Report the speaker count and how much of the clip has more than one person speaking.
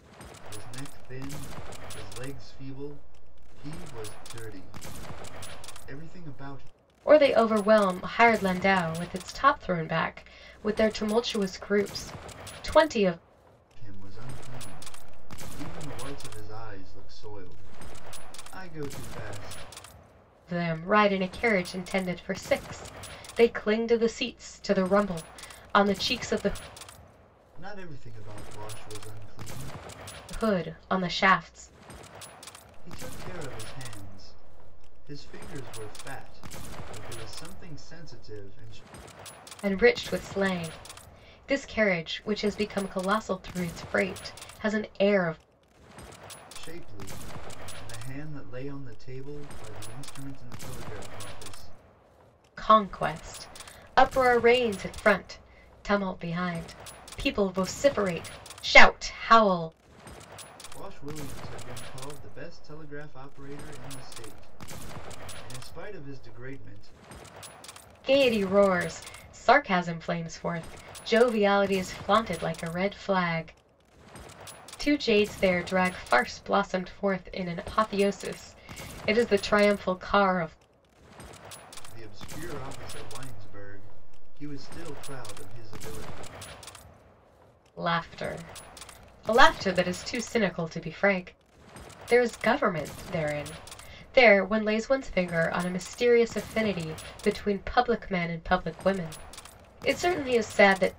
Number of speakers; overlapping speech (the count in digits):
2, no overlap